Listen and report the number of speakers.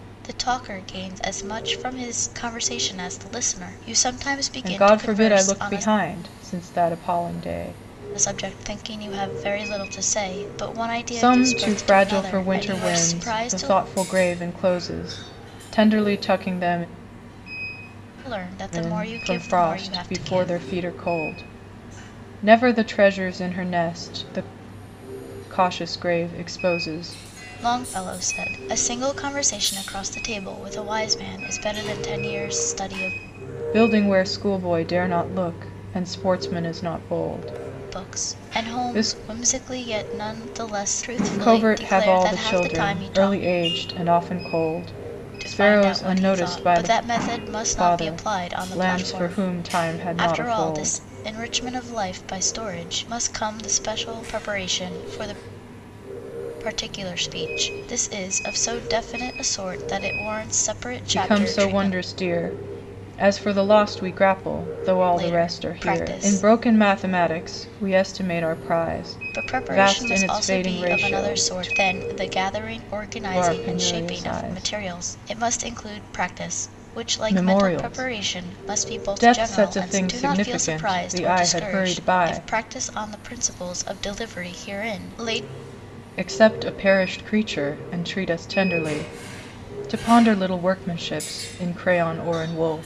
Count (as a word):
two